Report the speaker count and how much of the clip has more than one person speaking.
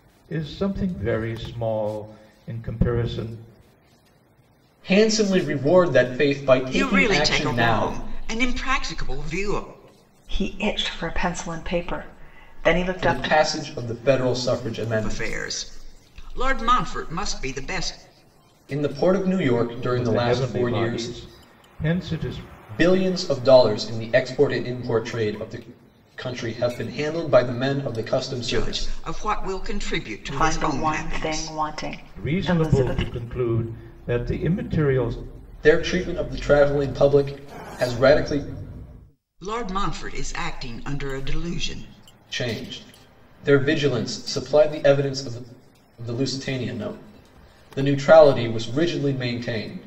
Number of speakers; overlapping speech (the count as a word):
four, about 12%